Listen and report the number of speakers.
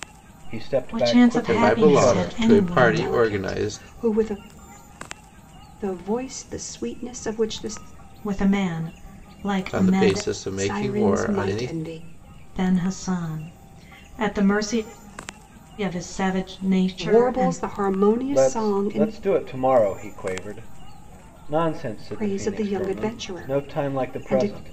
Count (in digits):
4